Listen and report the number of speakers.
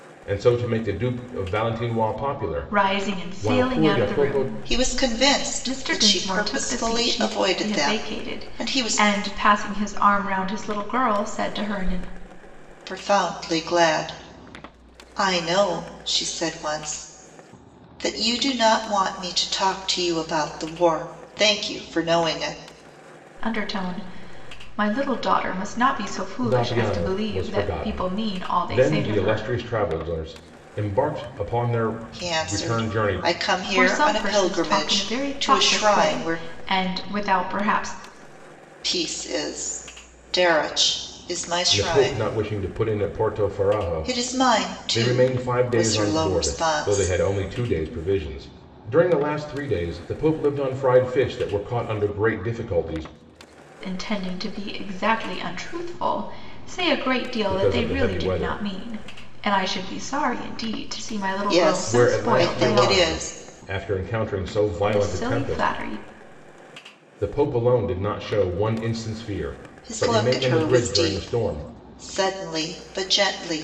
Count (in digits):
3